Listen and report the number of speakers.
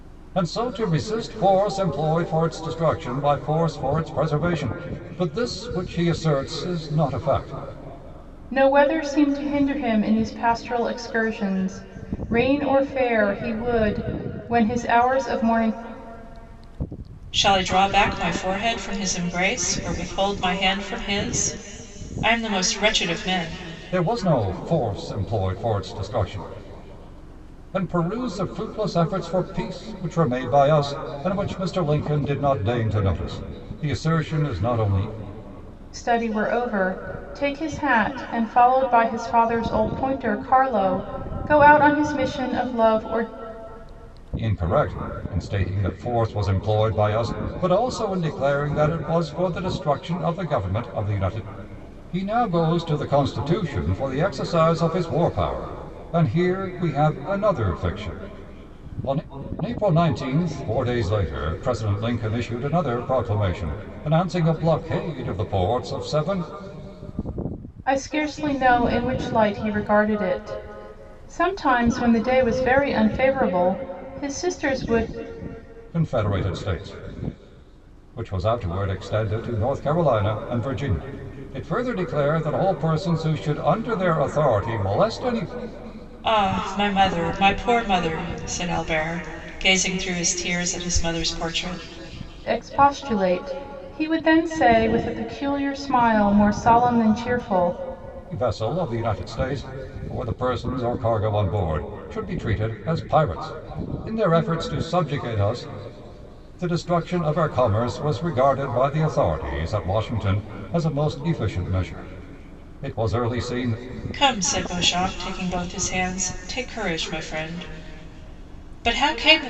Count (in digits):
3